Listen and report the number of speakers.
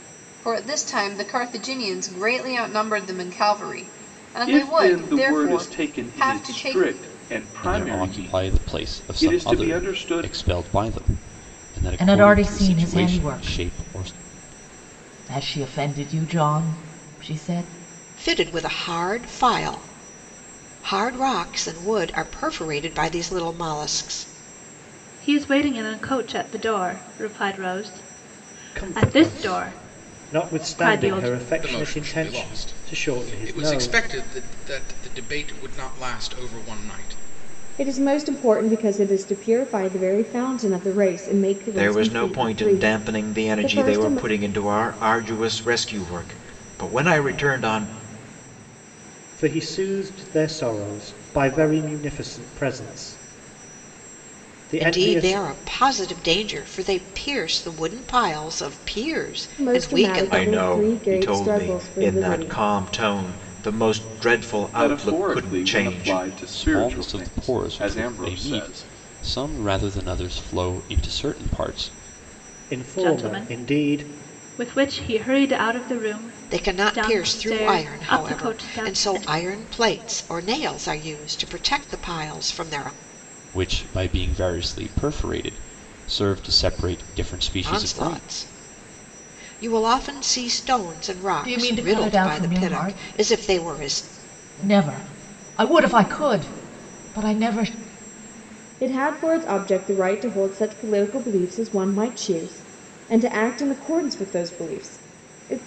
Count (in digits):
10